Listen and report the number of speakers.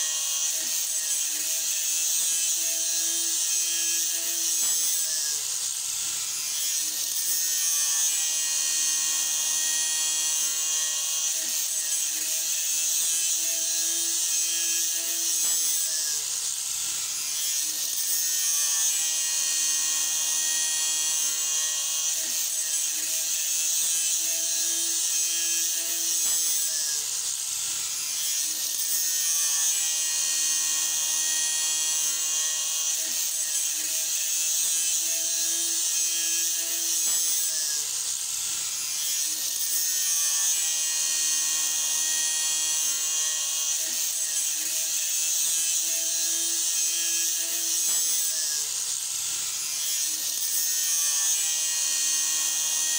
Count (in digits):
0